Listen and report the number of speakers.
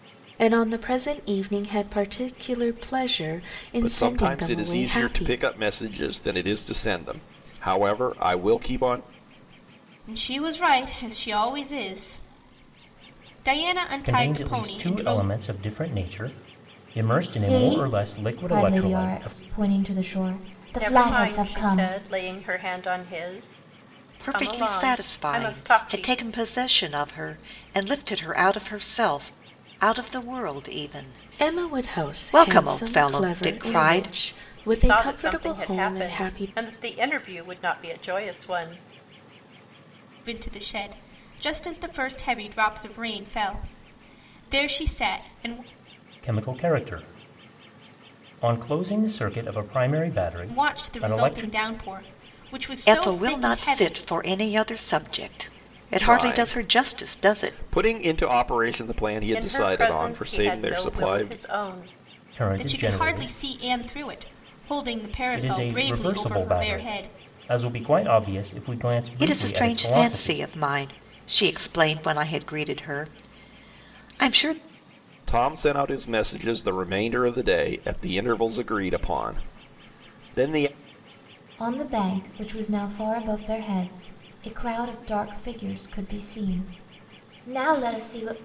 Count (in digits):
7